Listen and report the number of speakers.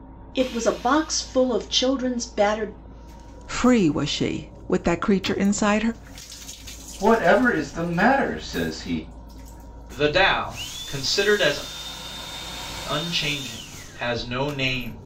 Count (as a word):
four